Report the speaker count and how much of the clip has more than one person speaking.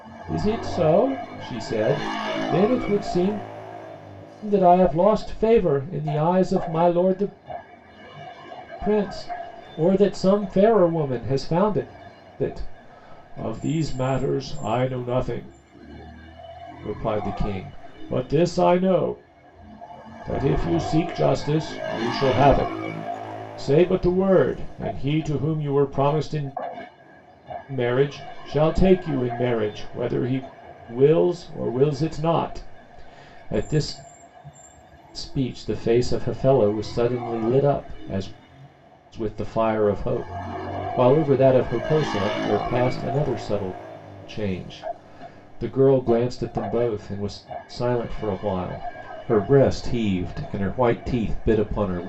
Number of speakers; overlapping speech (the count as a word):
one, no overlap